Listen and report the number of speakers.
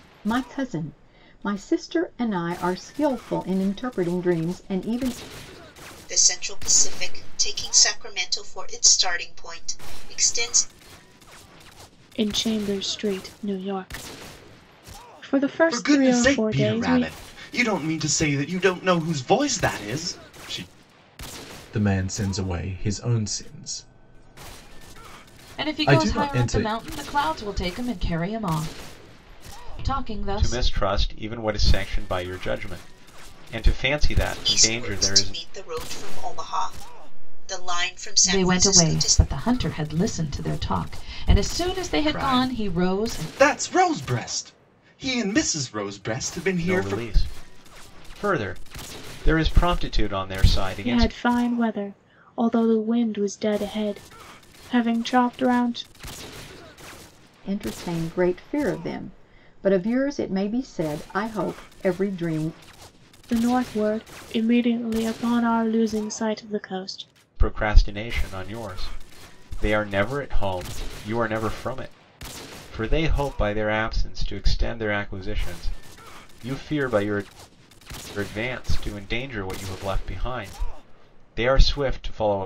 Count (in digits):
7